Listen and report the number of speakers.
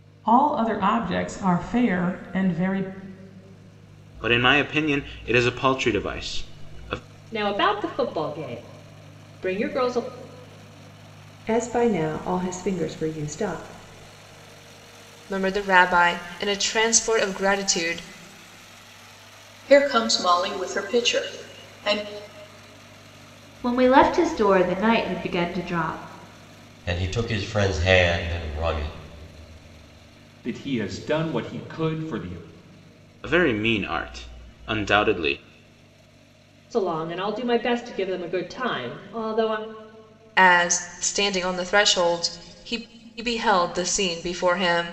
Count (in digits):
9